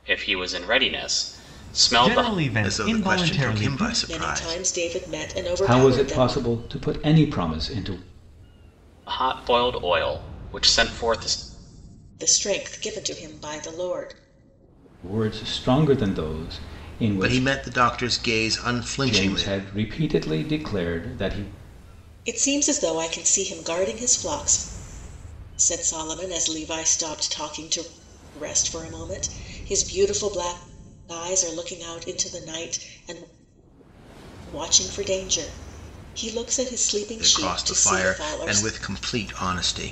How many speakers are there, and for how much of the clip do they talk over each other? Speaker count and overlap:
5, about 14%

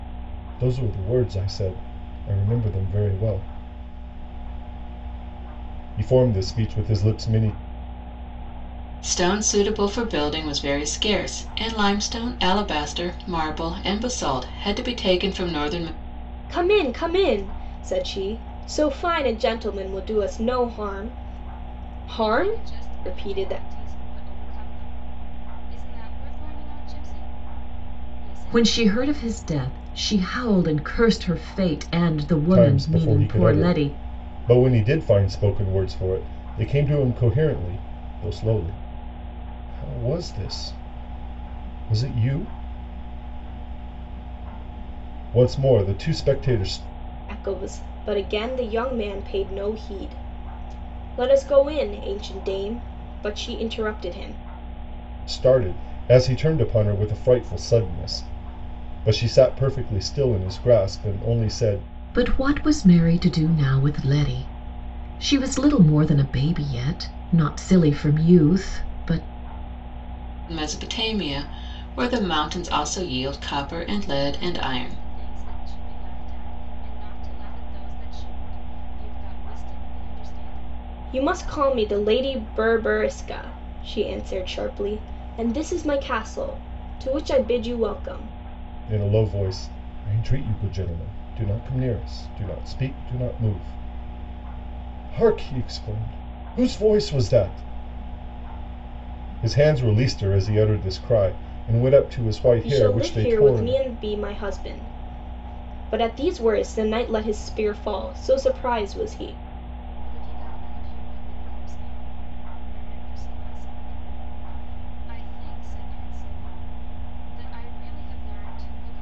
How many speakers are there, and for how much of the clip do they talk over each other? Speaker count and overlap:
5, about 5%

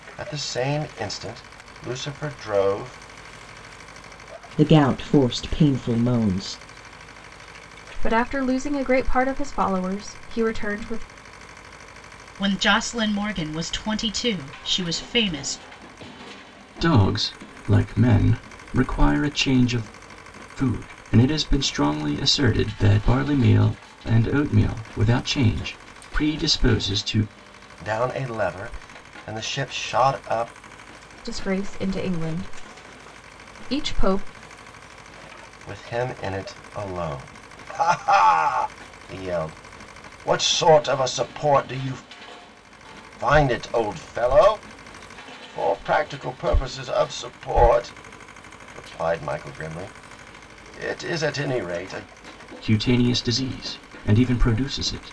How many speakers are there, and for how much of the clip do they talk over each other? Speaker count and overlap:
5, no overlap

